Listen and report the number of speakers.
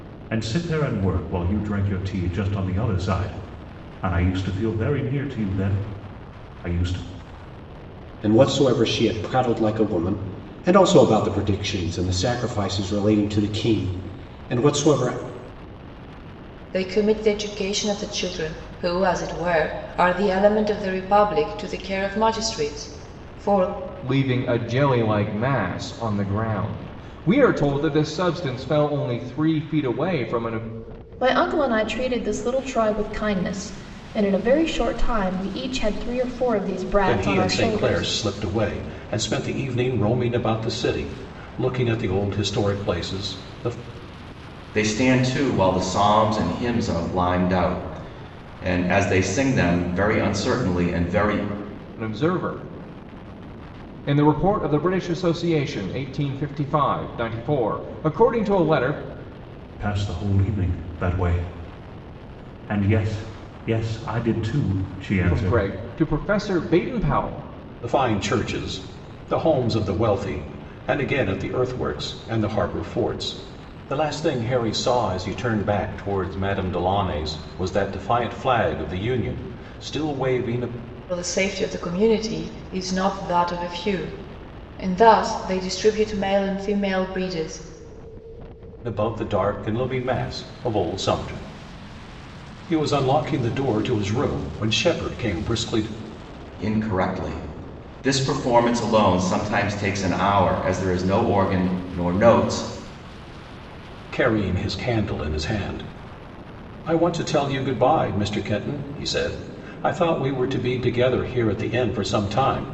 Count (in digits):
7